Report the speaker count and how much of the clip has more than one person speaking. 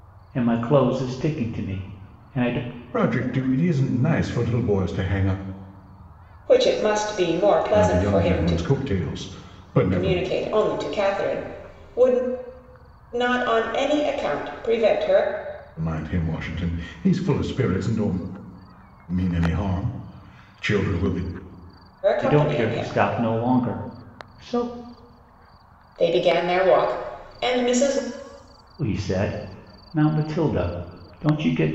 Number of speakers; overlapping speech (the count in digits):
3, about 6%